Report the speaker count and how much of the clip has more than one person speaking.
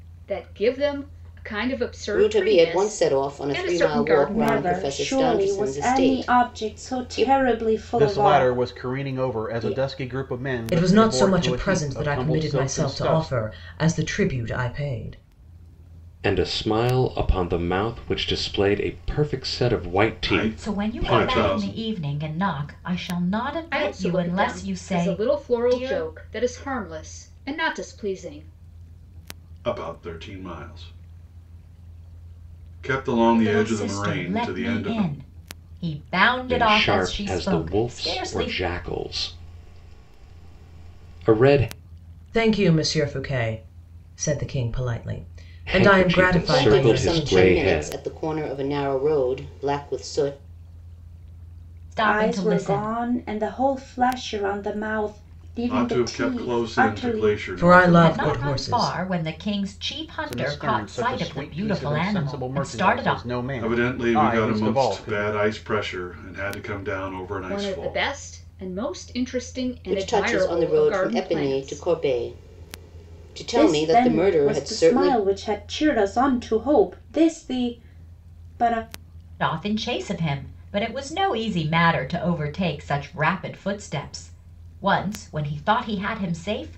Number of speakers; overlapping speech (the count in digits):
8, about 38%